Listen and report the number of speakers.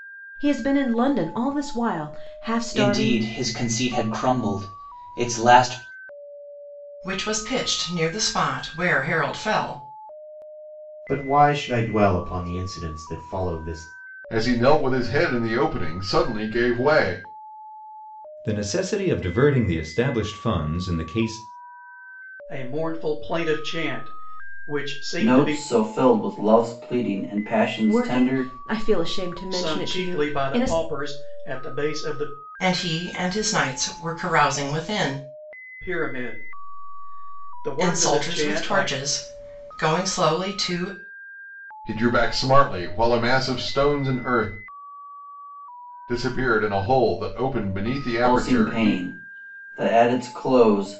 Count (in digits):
8